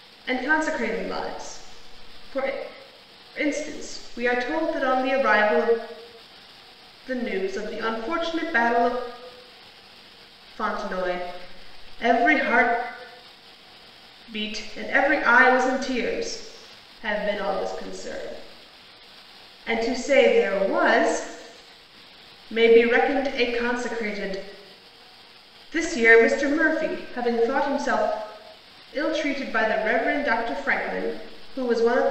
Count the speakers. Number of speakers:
1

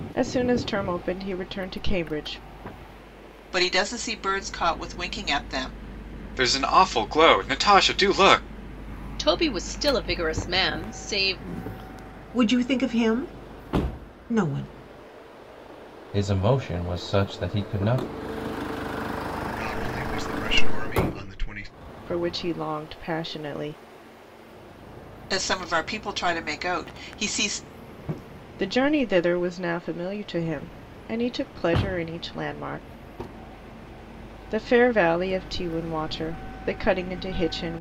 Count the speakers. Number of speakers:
7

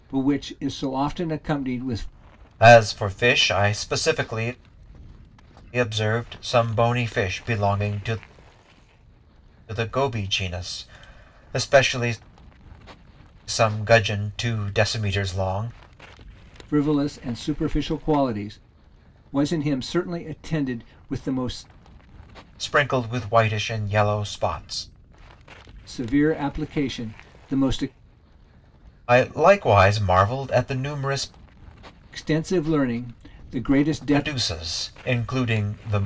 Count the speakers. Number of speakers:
2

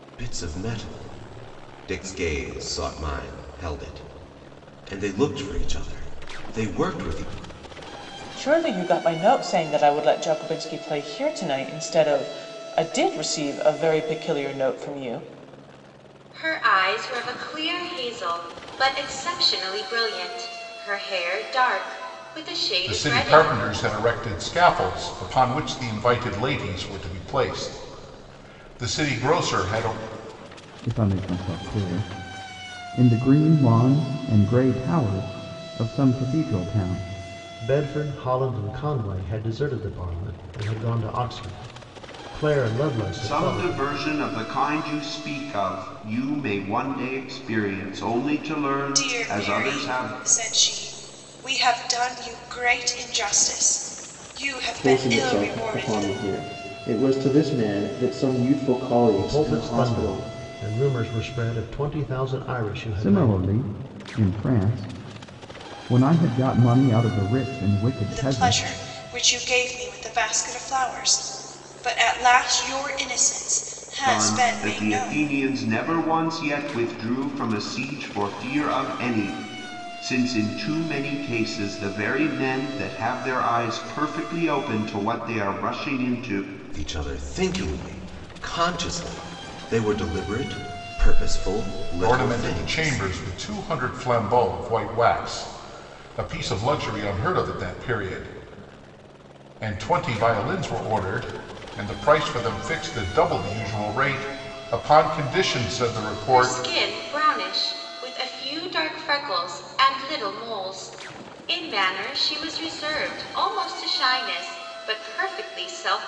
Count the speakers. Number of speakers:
9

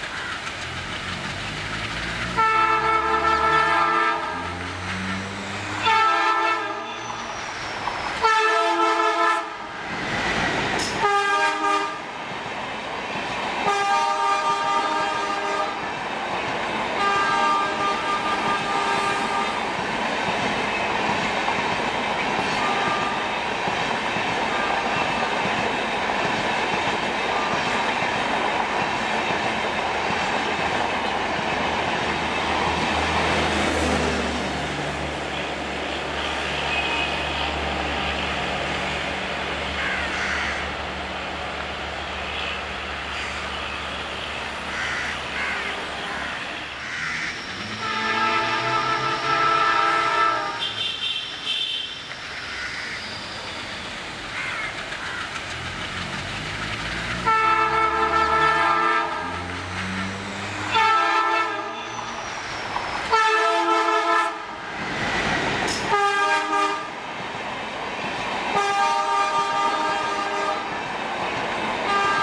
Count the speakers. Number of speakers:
0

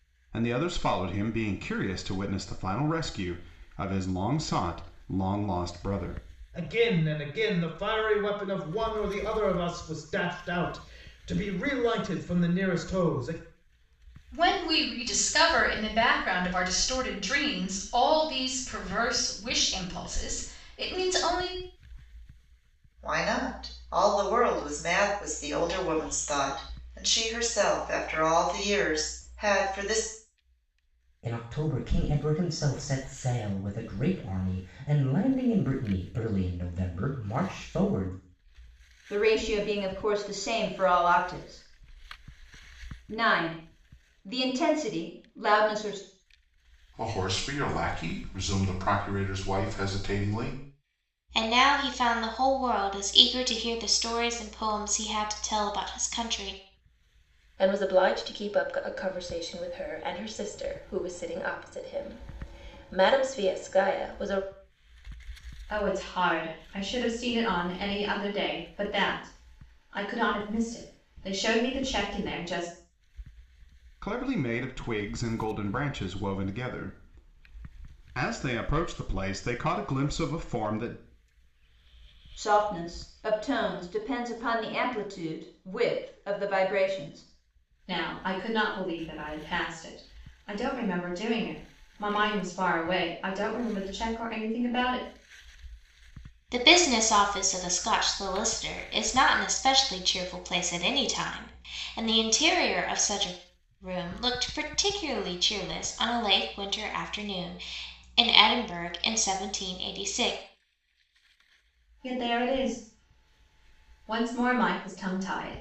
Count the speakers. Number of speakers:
10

